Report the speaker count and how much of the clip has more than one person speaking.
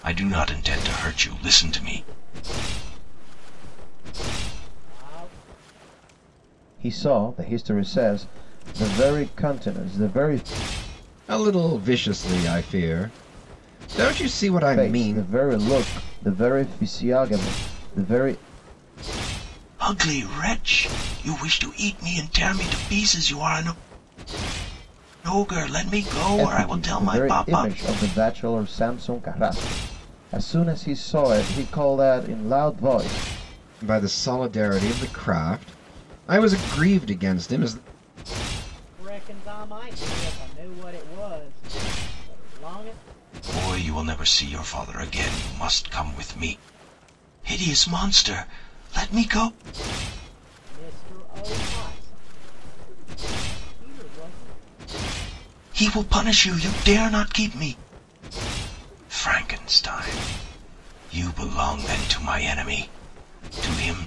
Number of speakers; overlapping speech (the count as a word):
four, about 4%